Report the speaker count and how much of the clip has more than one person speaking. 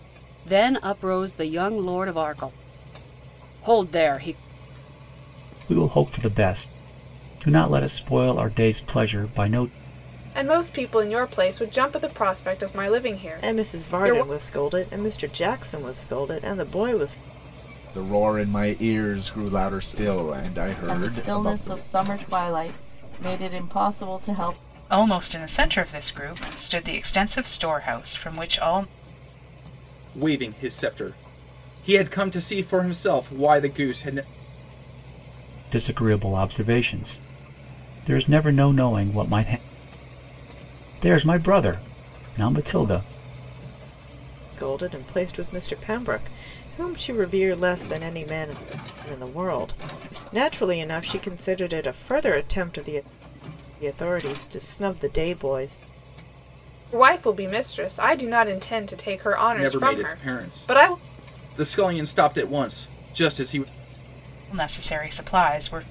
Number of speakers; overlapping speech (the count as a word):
eight, about 5%